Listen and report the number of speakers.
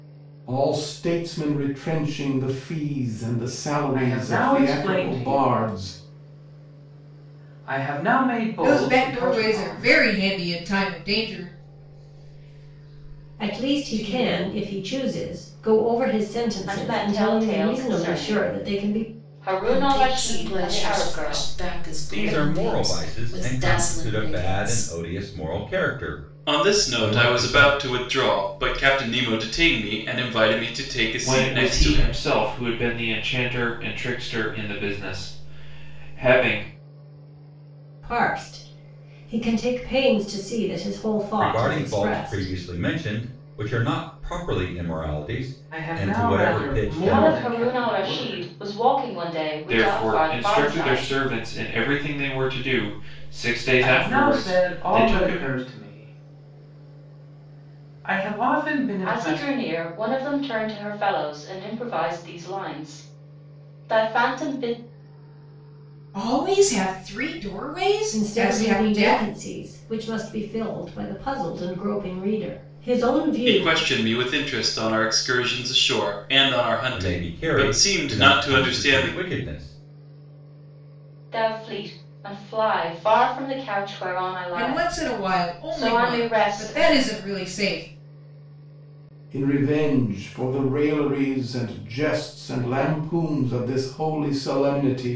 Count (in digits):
9